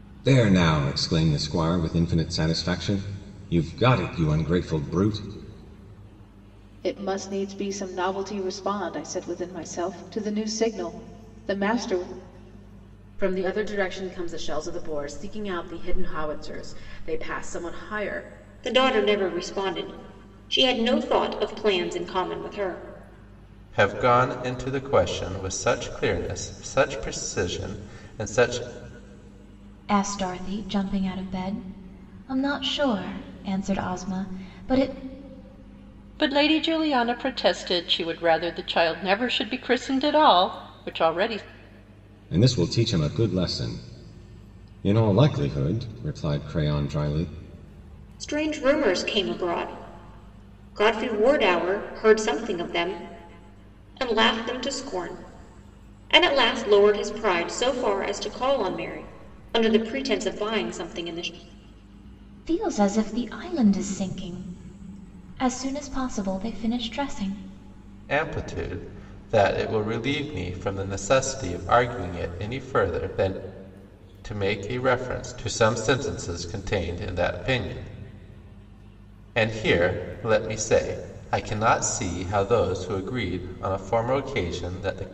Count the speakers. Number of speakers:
7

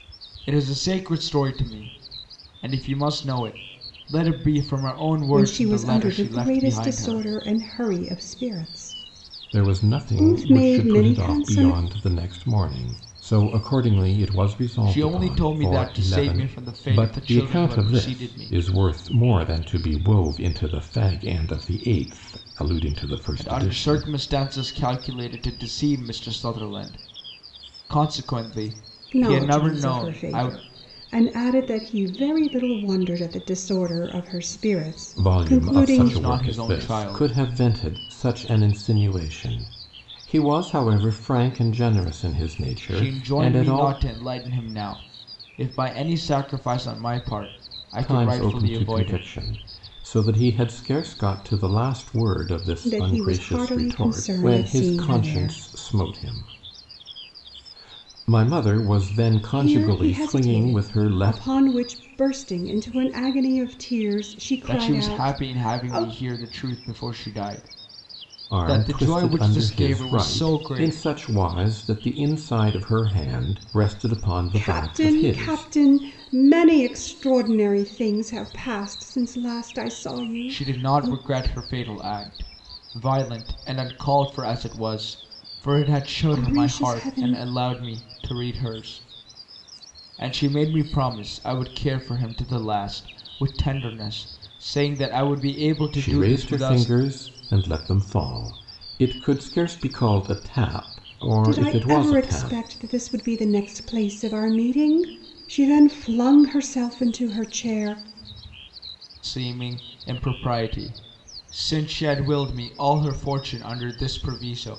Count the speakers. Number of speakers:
3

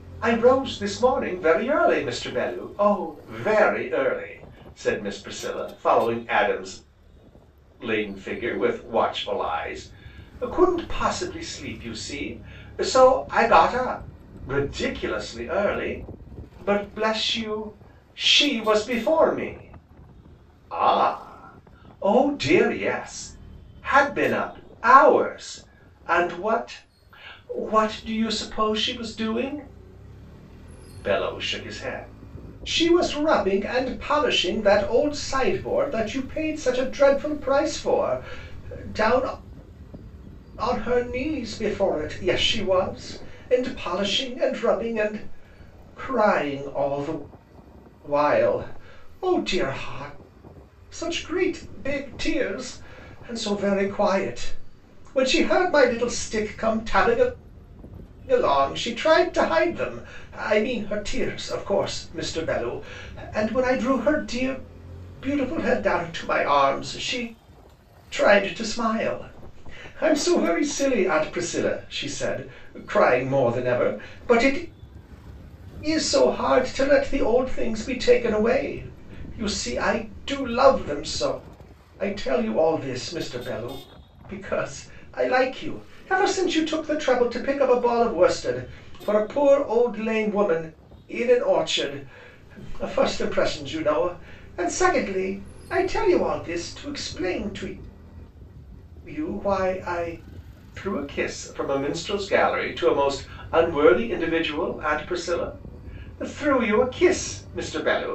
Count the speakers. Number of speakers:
1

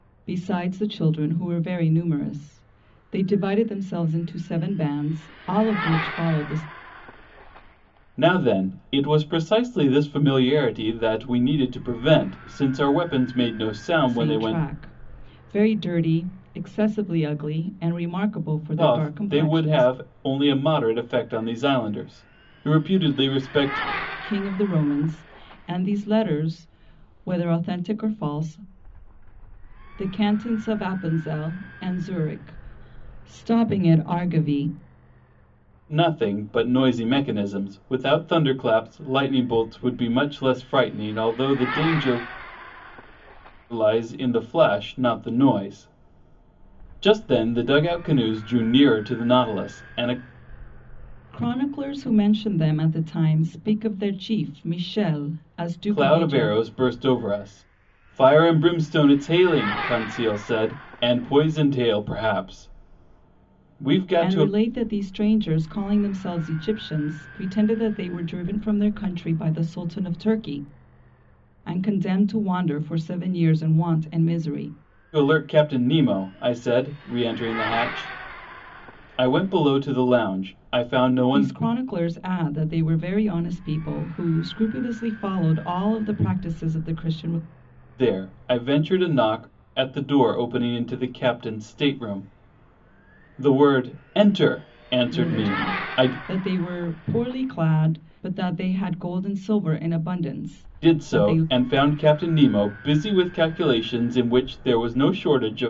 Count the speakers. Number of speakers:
2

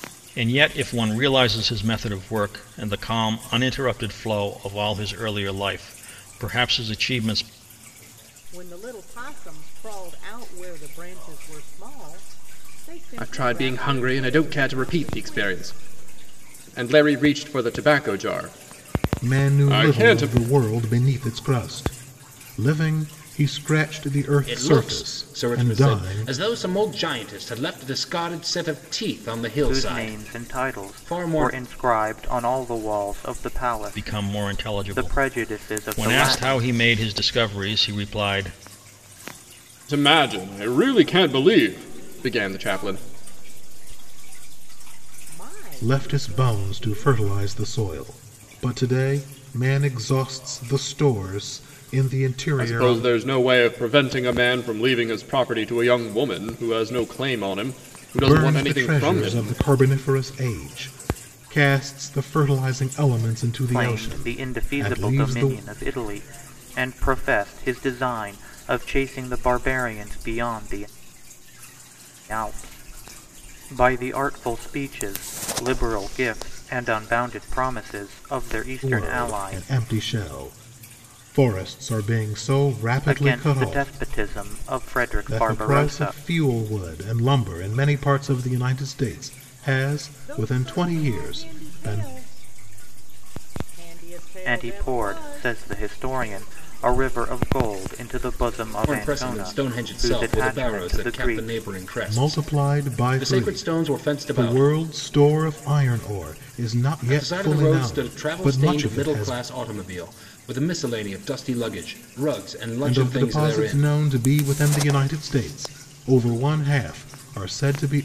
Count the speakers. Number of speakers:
6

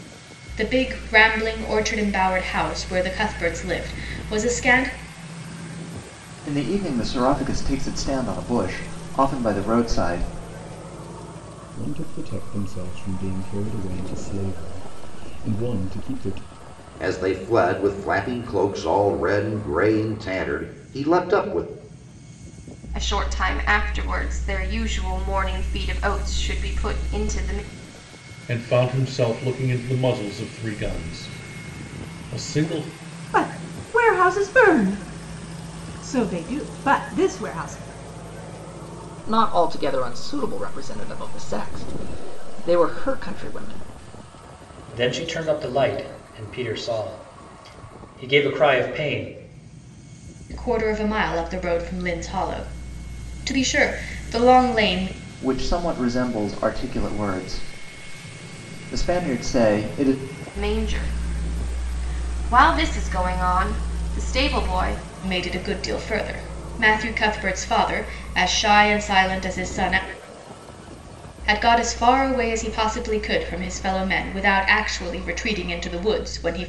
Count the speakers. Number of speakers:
9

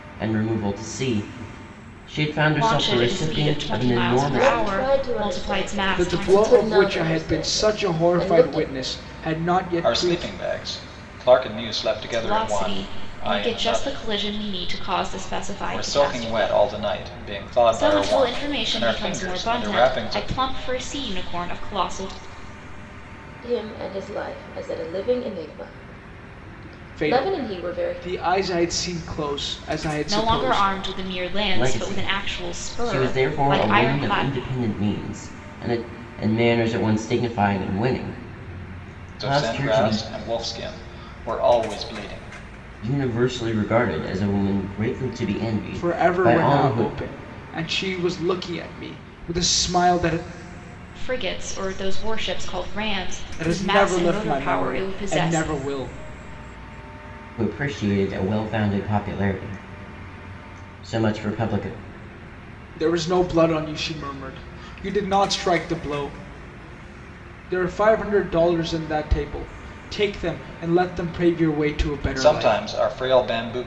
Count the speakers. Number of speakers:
5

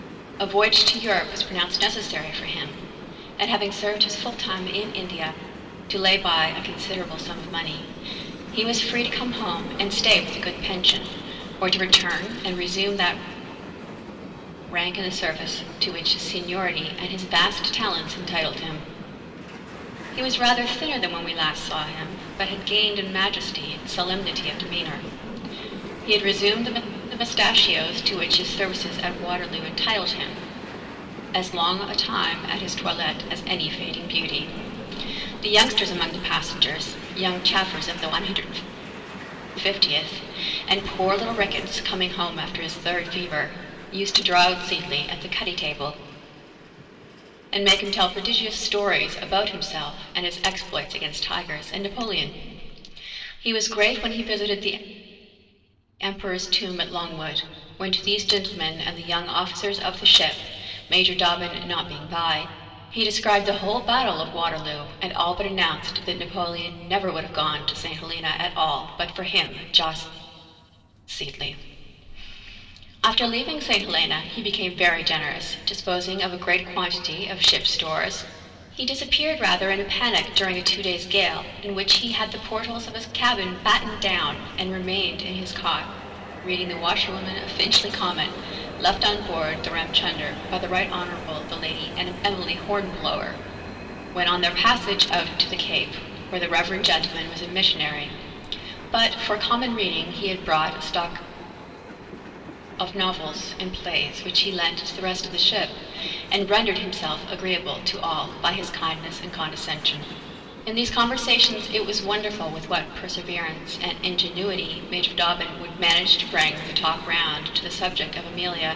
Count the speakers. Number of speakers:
1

